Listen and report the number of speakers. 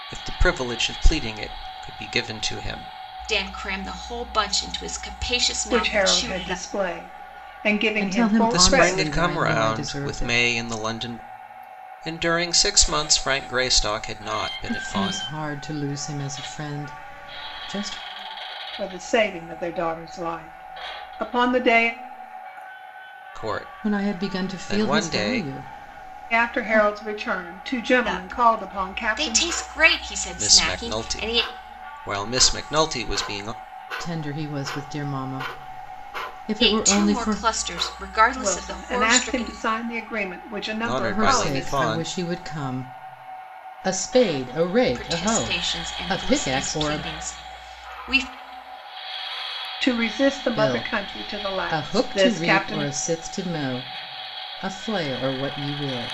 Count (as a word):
four